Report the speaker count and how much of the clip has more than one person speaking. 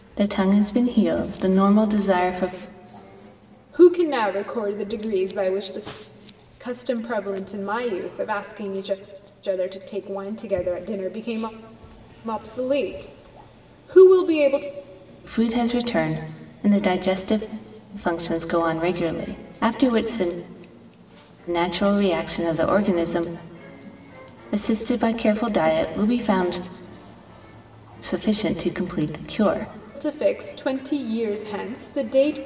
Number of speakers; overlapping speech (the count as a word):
two, no overlap